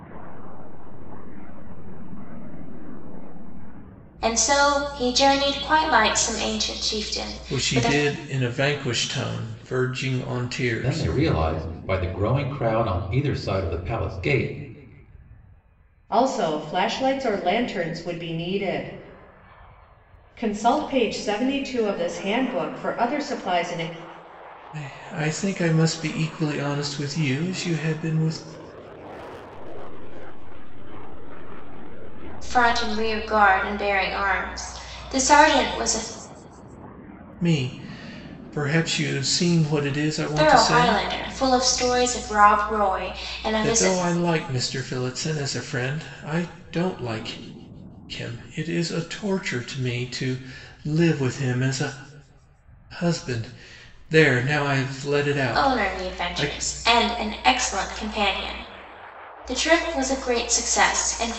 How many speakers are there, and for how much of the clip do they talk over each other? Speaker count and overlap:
five, about 6%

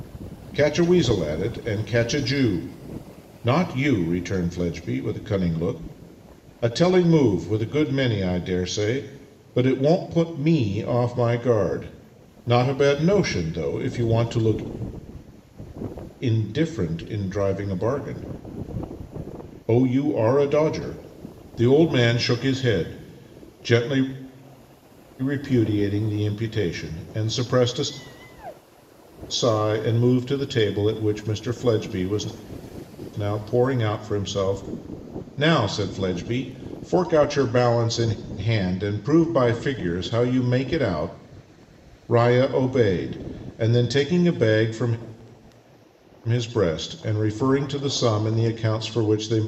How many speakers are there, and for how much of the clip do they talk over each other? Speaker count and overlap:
one, no overlap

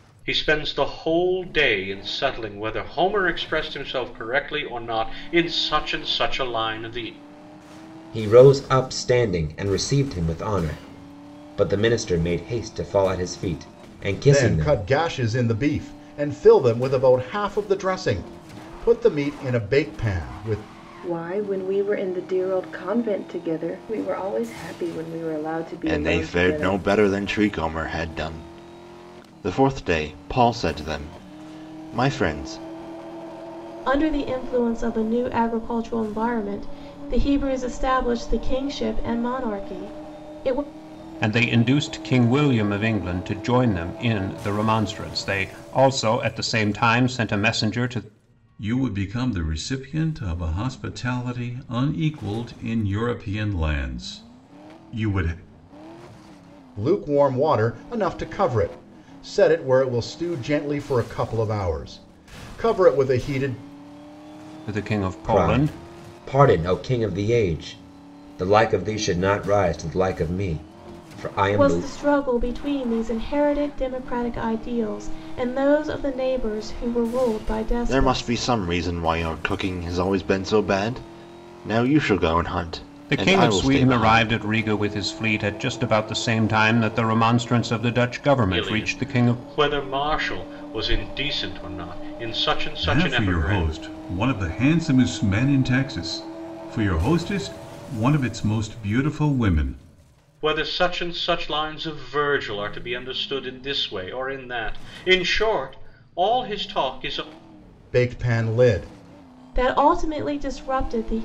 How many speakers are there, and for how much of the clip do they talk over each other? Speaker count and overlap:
eight, about 6%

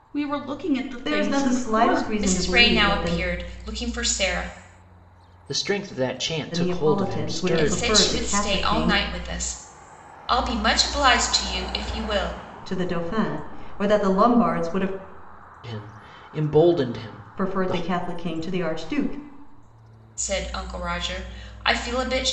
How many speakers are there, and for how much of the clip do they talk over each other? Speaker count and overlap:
four, about 24%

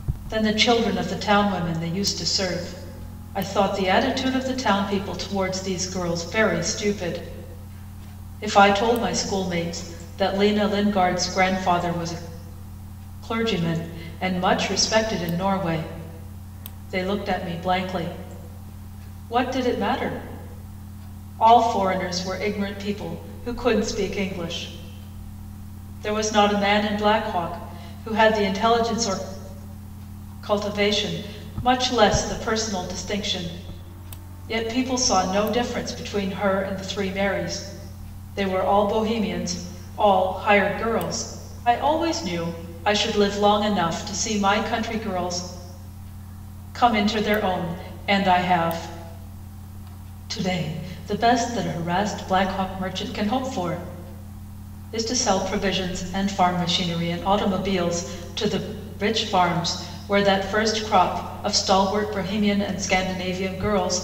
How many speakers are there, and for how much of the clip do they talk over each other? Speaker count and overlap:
one, no overlap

